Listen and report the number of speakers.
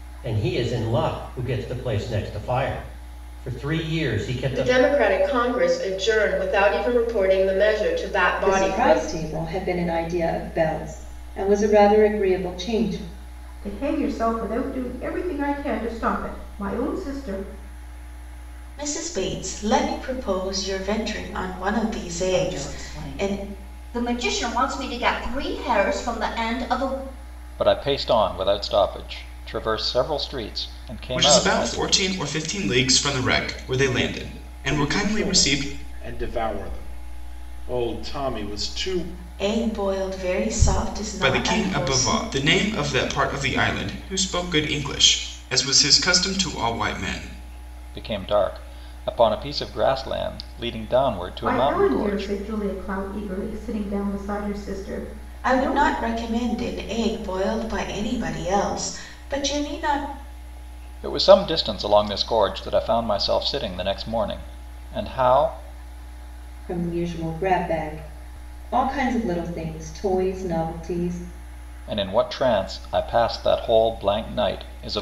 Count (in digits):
9